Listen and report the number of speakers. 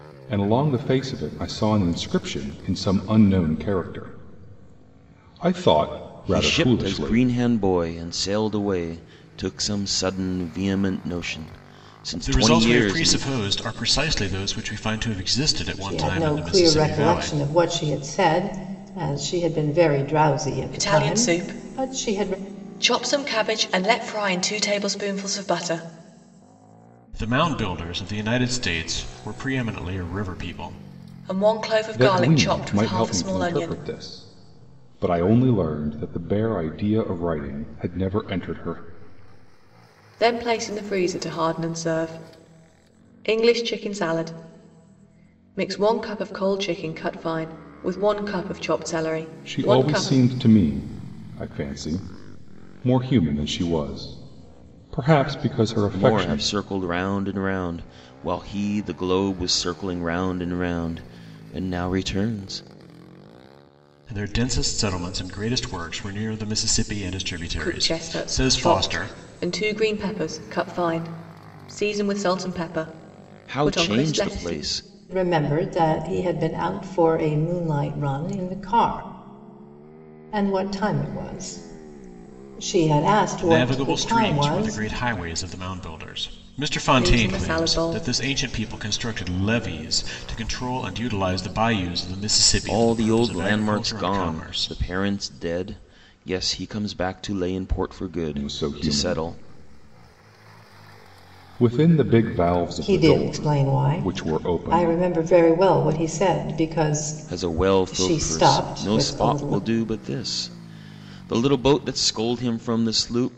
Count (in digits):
5